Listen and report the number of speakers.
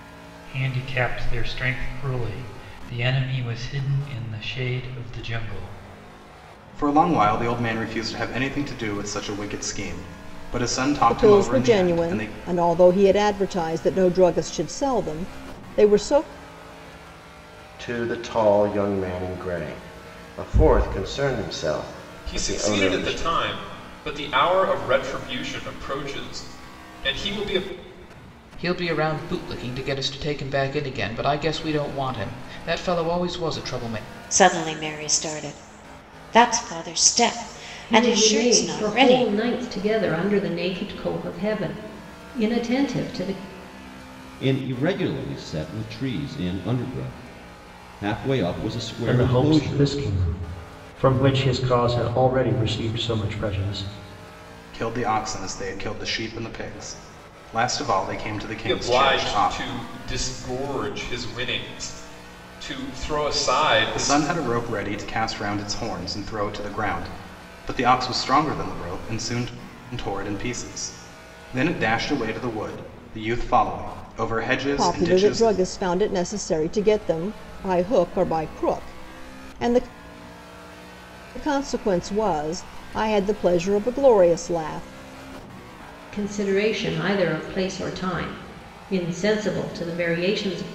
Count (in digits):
10